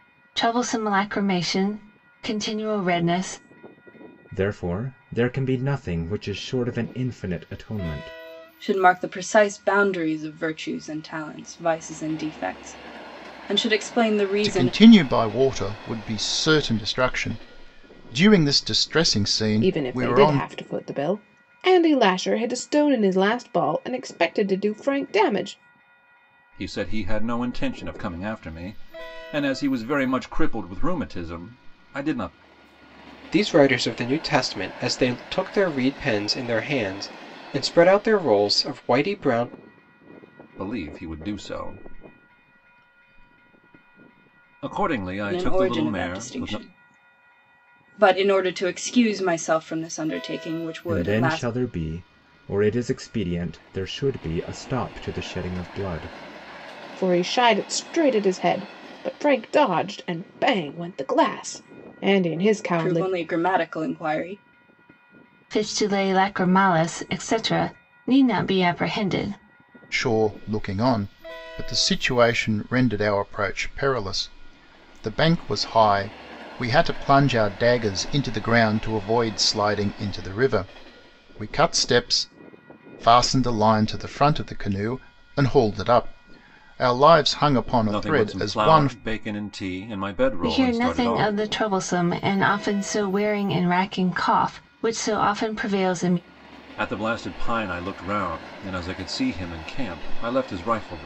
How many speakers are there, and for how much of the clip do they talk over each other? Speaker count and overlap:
seven, about 6%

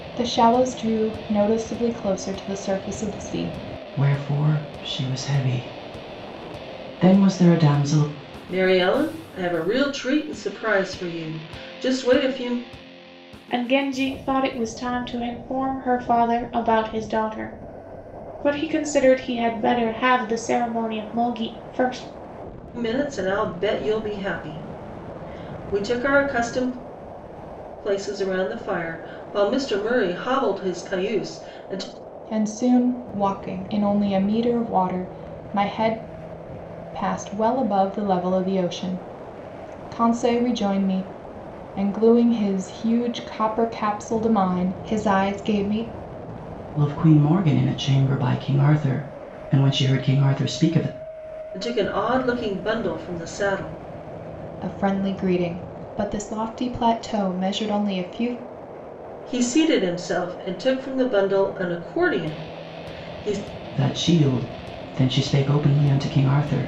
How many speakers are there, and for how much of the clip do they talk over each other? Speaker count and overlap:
four, no overlap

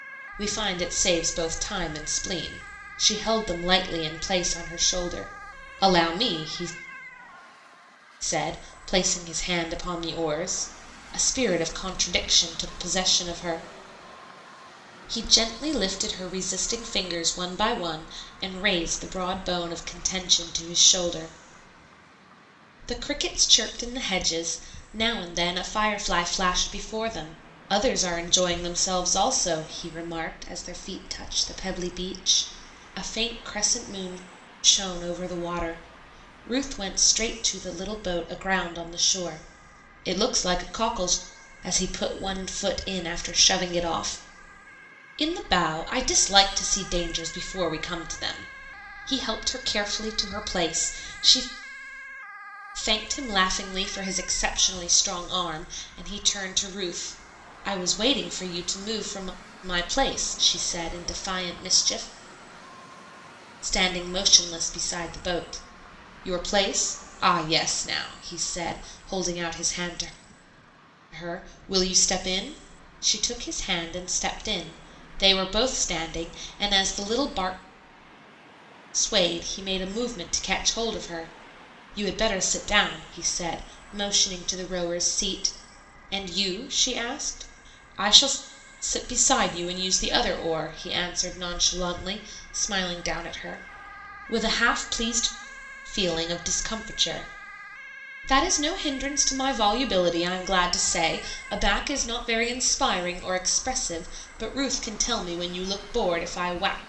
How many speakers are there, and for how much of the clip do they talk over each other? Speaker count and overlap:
one, no overlap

